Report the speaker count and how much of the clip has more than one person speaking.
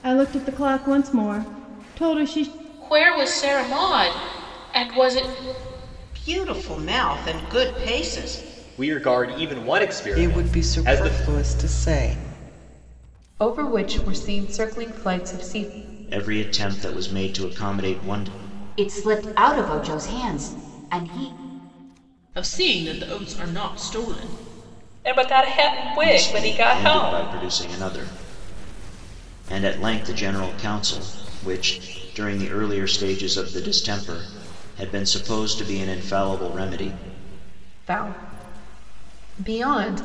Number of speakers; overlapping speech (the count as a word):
ten, about 6%